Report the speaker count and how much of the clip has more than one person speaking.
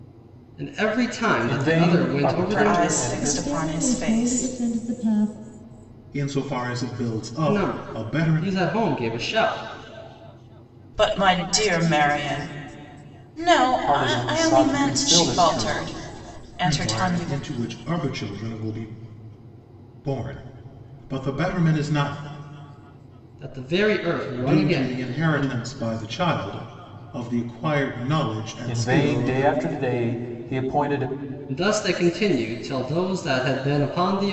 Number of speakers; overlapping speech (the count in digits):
5, about 26%